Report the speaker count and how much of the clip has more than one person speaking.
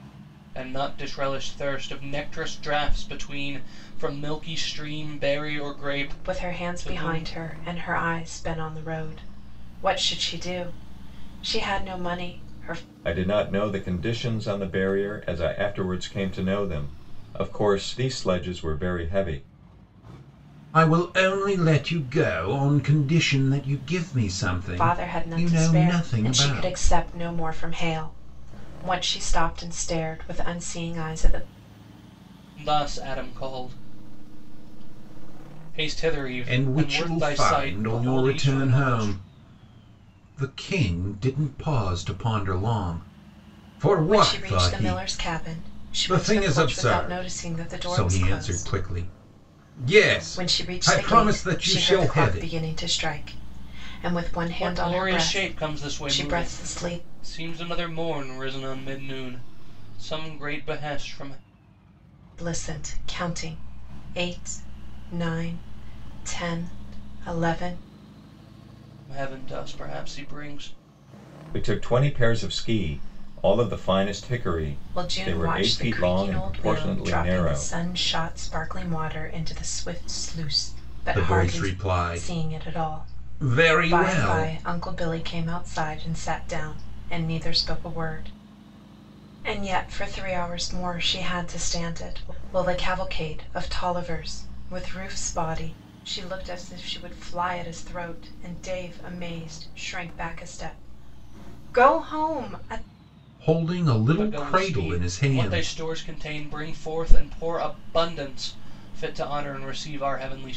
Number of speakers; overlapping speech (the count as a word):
four, about 20%